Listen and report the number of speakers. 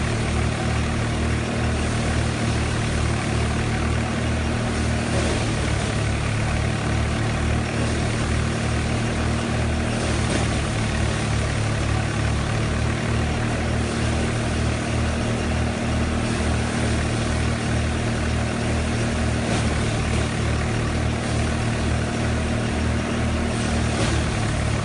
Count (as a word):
zero